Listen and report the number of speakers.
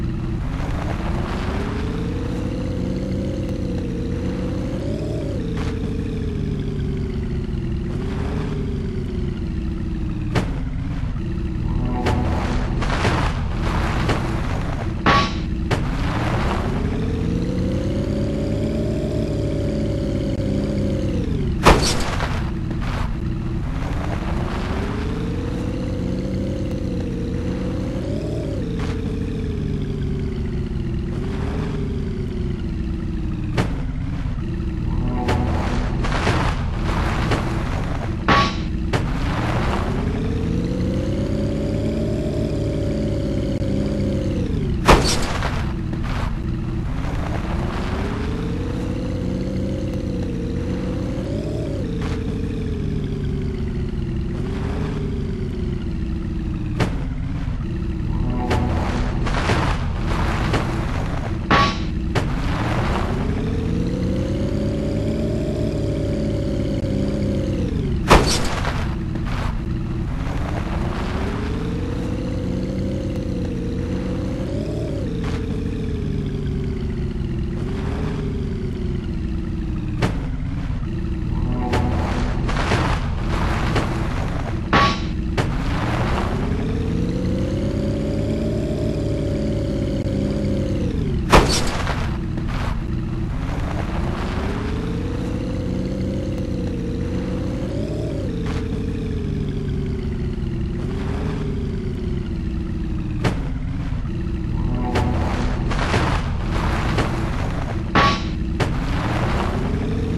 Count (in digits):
0